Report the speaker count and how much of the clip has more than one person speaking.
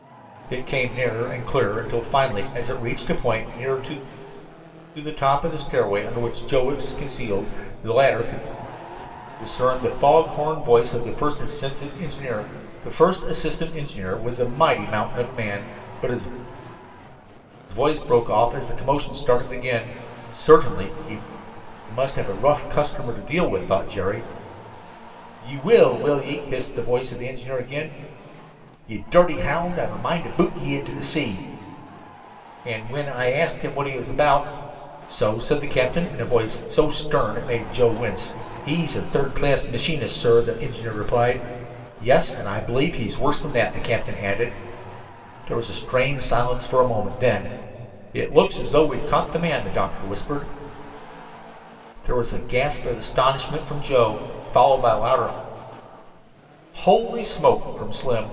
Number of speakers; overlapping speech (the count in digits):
1, no overlap